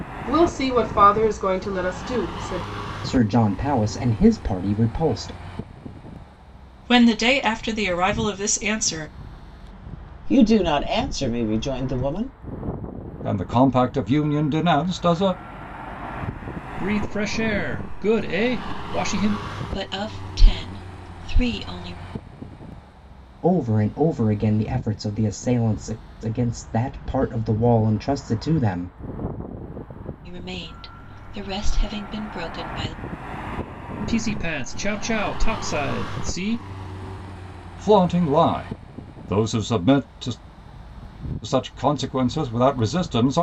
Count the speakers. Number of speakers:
7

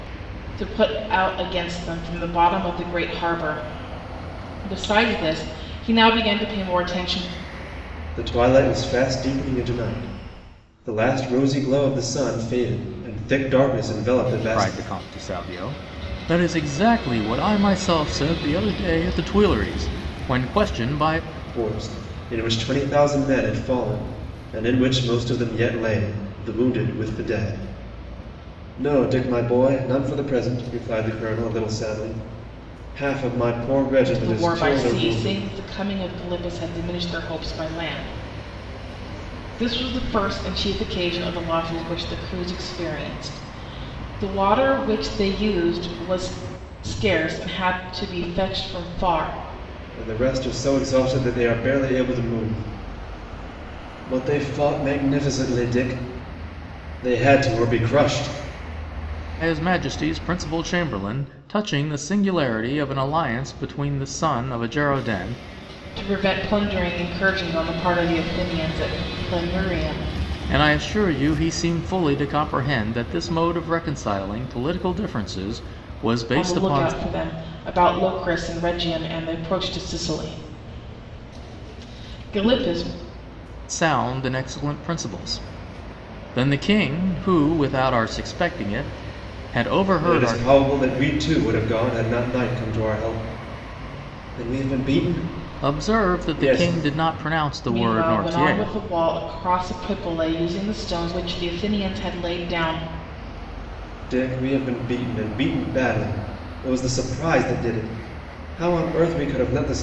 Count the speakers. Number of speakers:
3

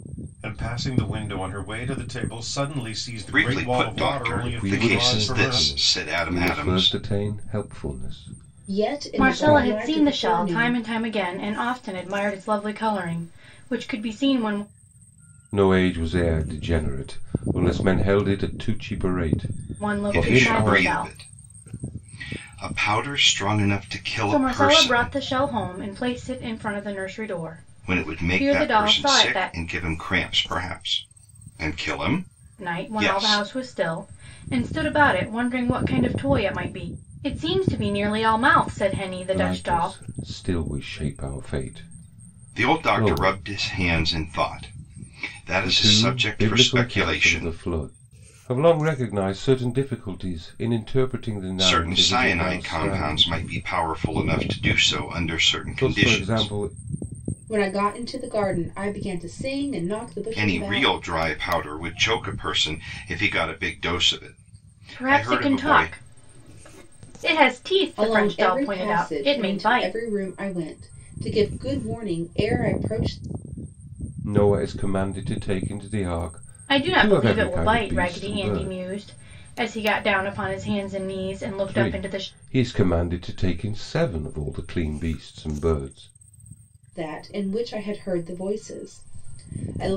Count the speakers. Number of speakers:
5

